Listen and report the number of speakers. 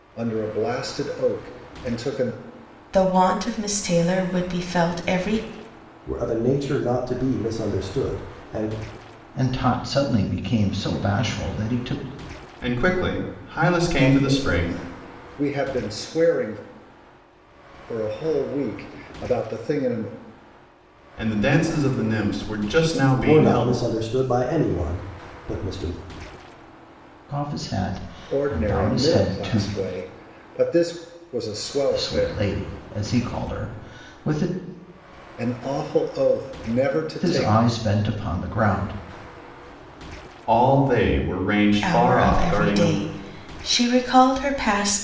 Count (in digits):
5